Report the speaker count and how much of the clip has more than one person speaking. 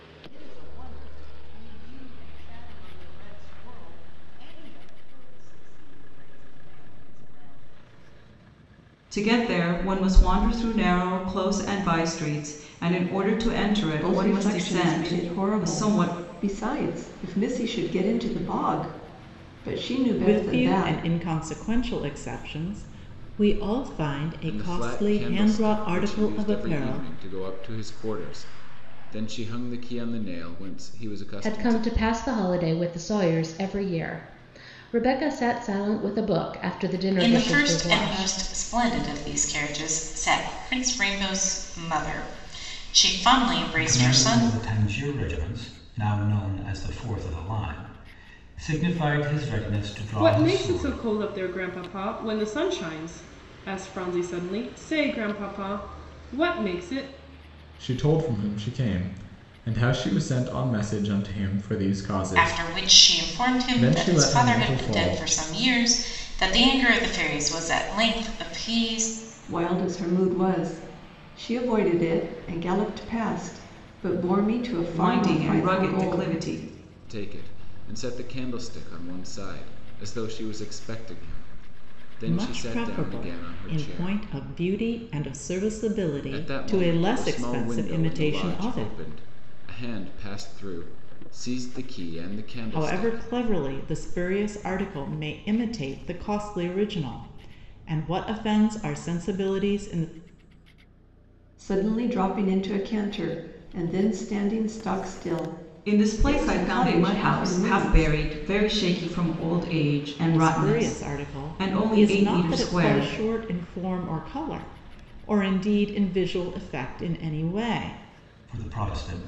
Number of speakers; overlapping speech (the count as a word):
ten, about 20%